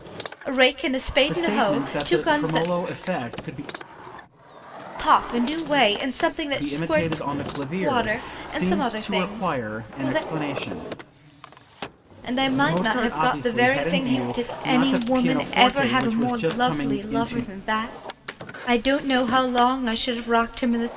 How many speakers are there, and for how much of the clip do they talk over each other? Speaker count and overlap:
2, about 46%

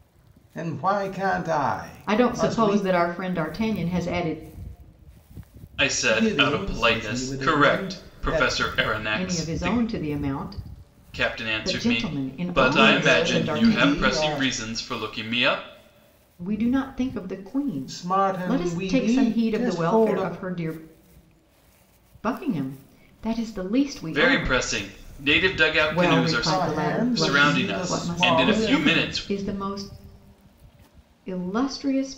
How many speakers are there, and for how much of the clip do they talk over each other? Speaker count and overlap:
3, about 41%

